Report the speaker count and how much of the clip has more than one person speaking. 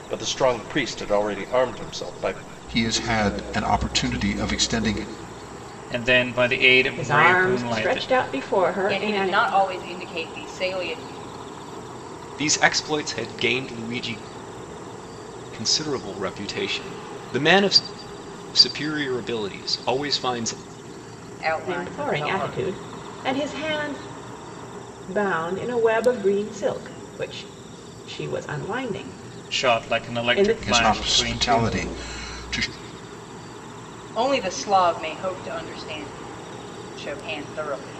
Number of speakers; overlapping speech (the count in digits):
6, about 13%